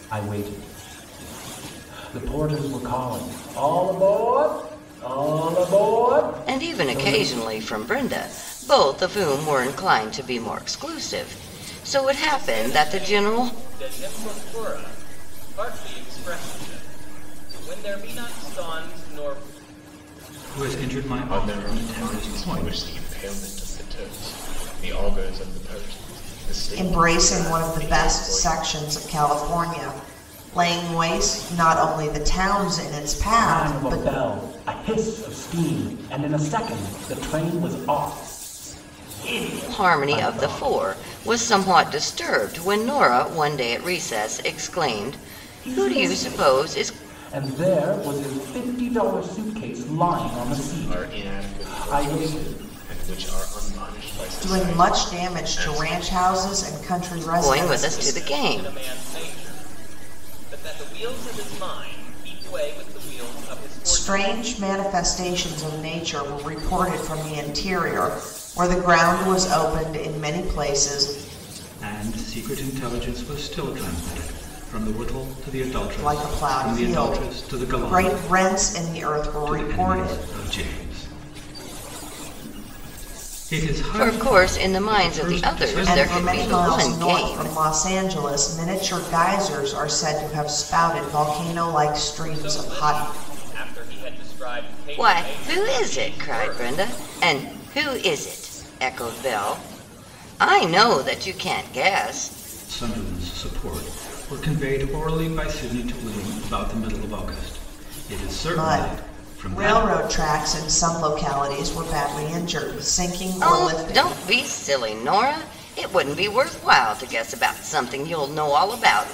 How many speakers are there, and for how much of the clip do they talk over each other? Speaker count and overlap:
six, about 23%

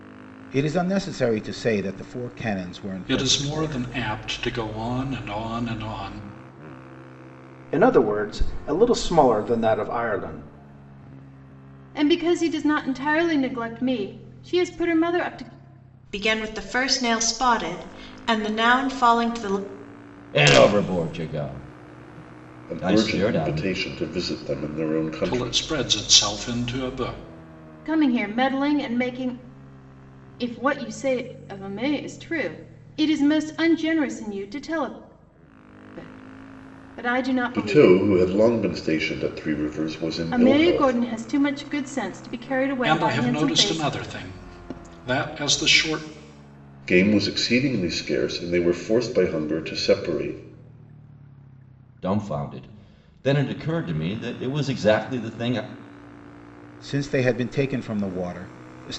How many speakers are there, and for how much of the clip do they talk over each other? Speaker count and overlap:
seven, about 8%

